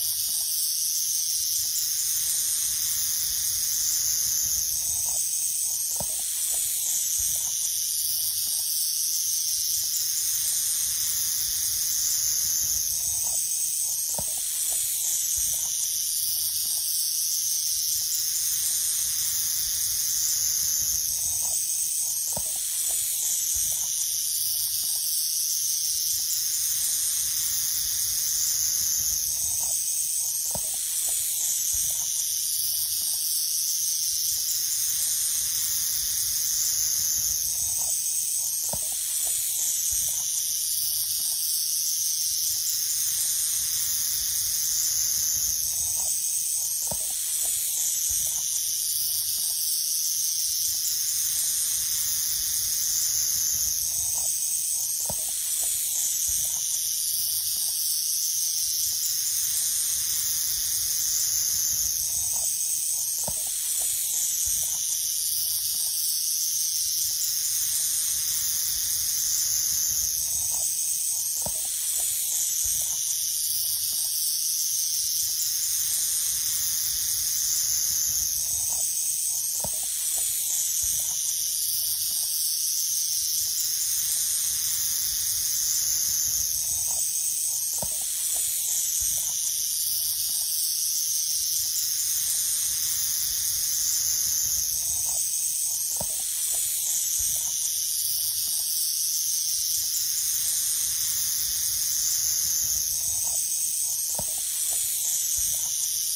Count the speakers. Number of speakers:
zero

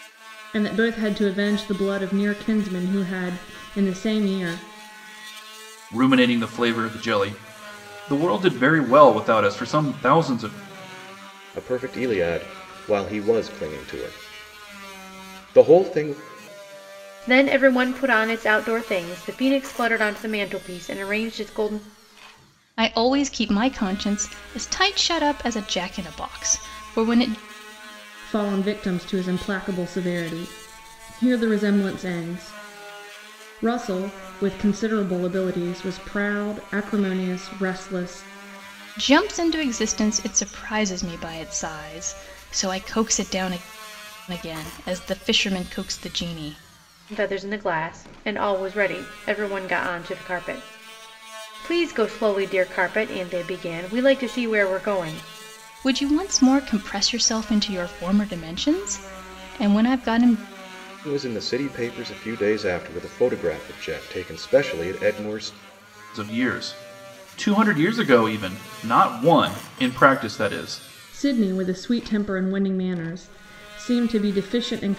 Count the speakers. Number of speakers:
five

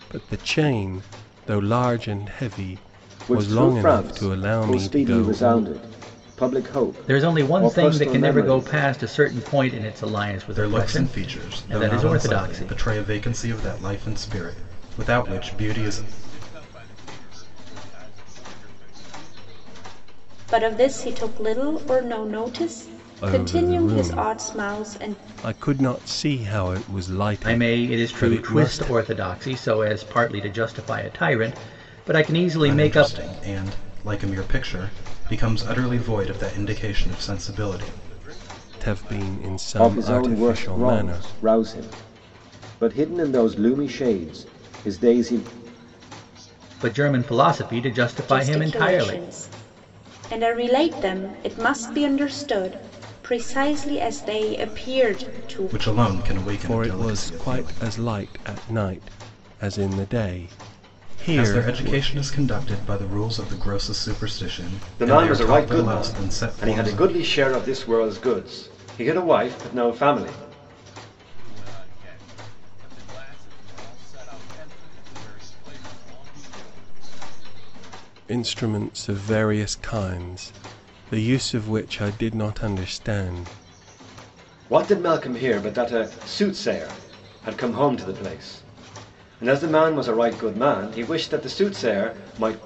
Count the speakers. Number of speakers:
six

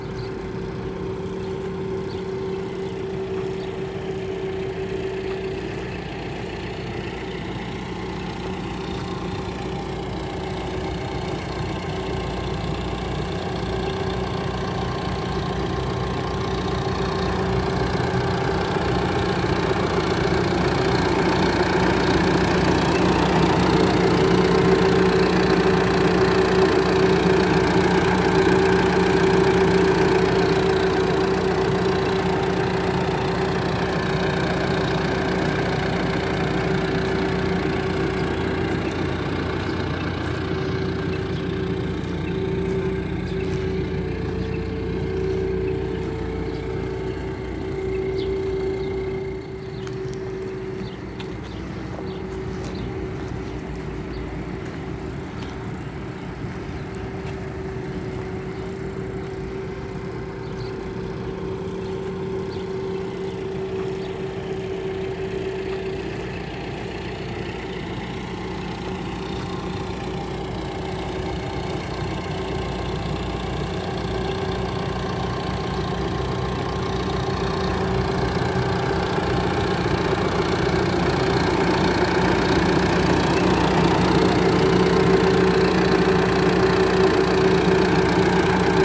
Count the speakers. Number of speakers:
zero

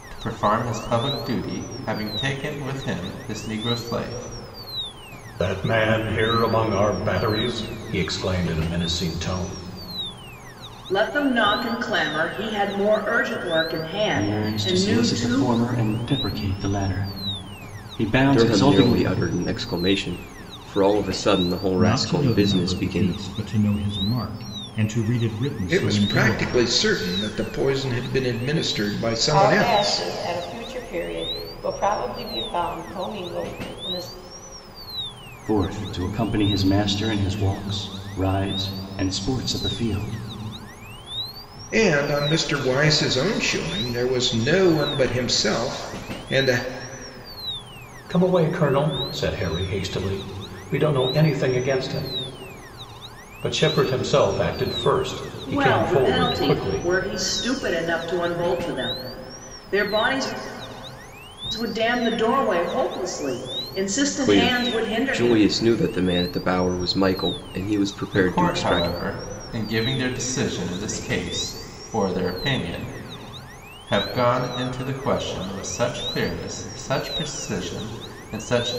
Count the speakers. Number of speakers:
eight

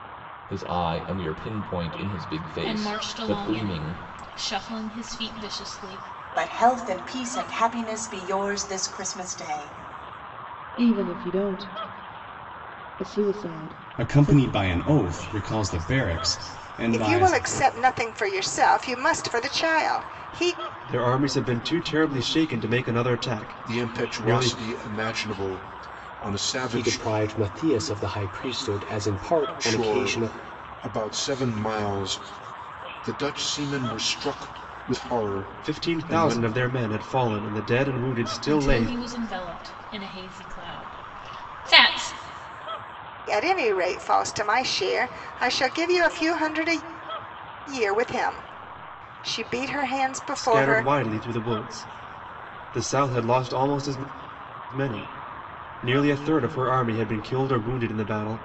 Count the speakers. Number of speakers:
nine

